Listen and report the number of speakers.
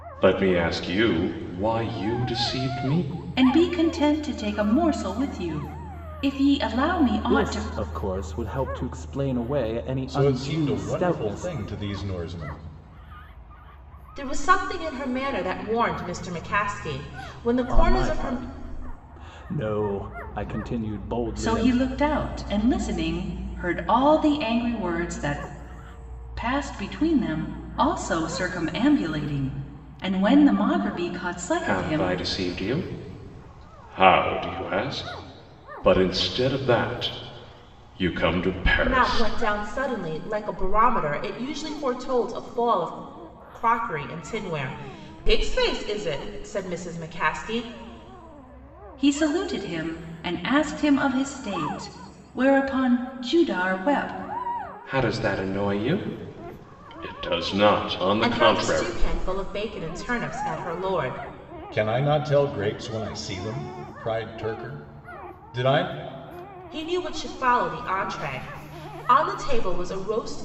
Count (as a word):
five